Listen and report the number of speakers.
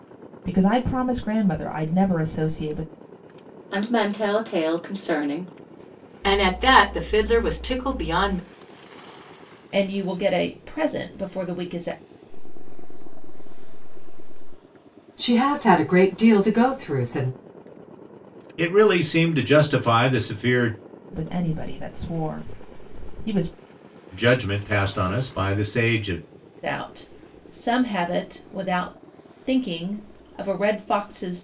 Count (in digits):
7